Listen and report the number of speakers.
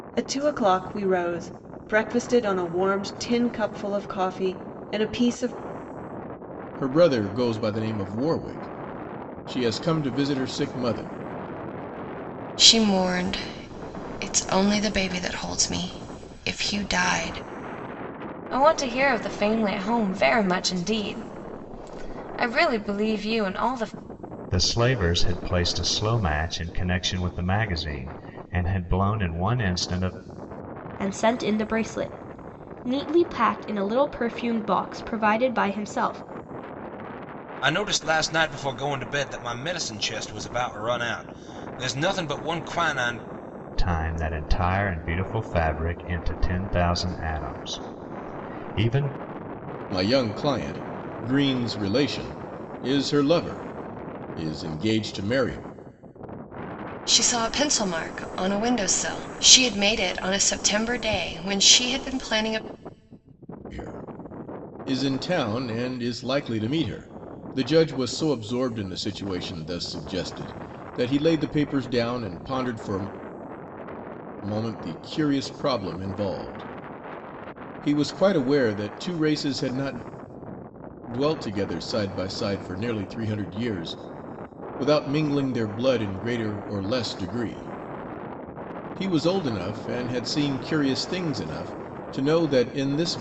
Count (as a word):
seven